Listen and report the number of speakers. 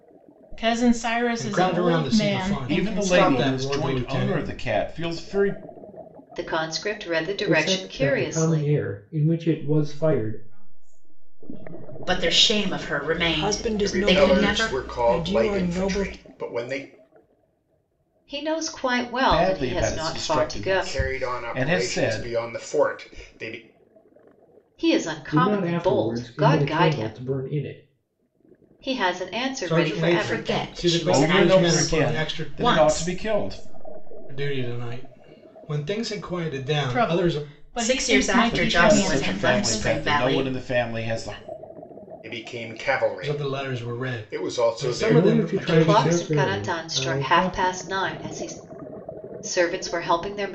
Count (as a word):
nine